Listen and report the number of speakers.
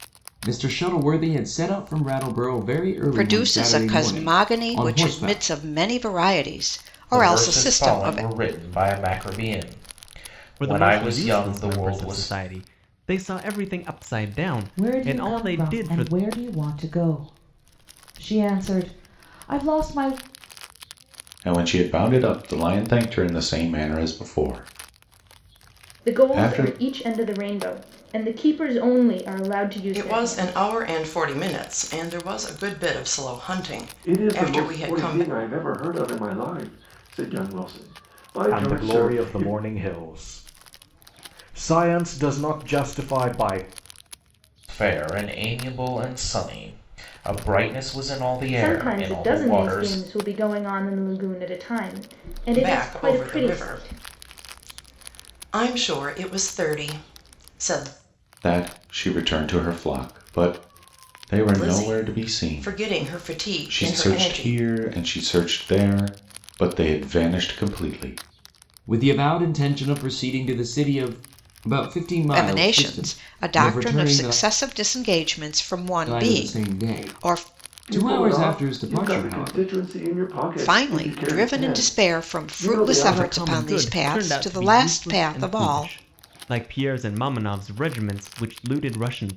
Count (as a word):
ten